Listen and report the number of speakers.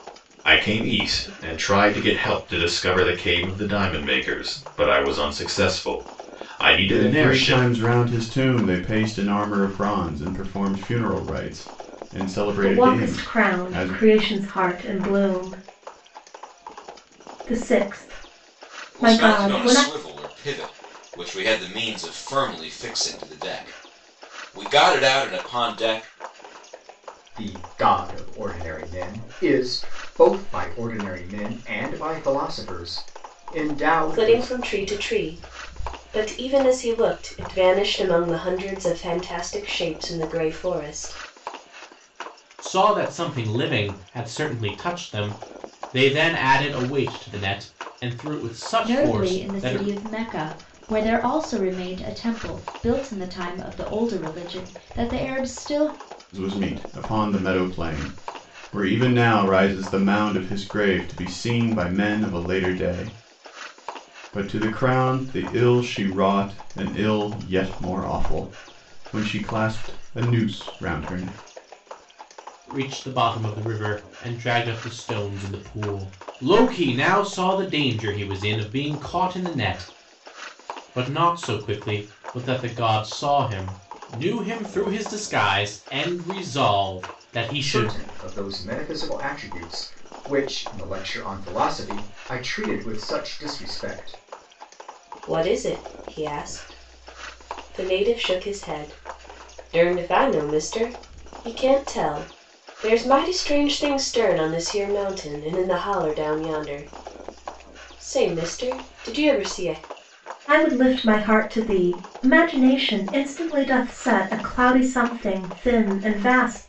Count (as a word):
eight